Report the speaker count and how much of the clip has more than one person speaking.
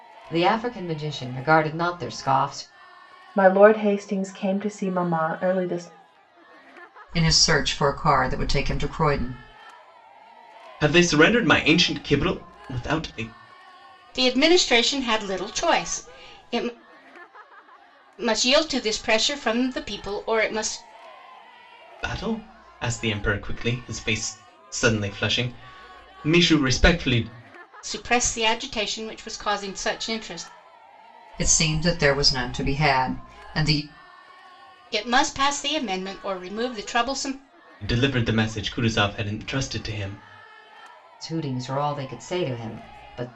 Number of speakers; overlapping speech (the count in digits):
5, no overlap